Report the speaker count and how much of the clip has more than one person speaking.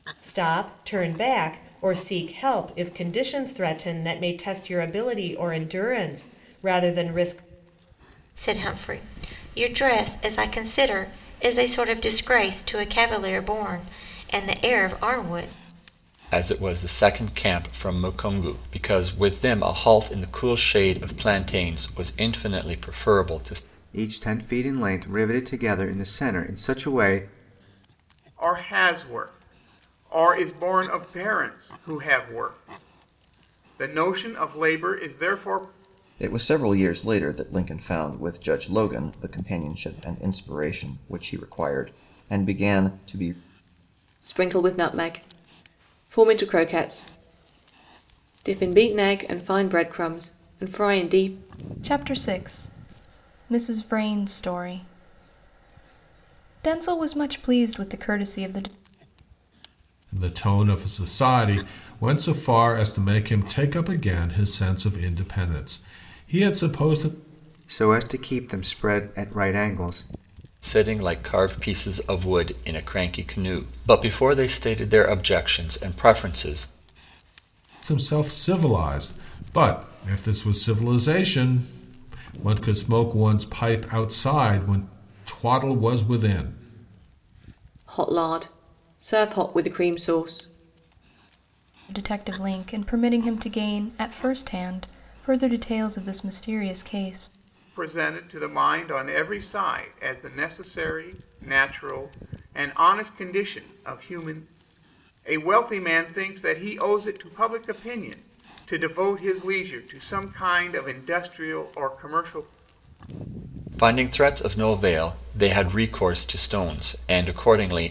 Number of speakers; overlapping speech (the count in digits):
9, no overlap